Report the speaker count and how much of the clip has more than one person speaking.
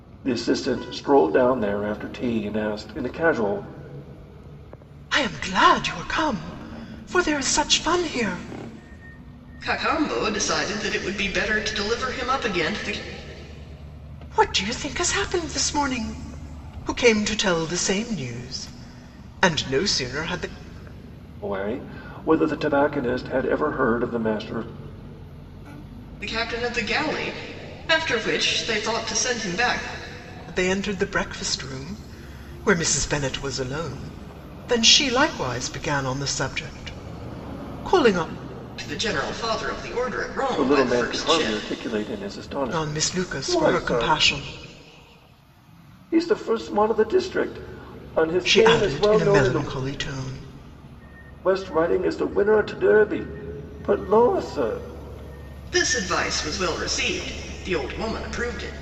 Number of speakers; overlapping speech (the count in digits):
3, about 7%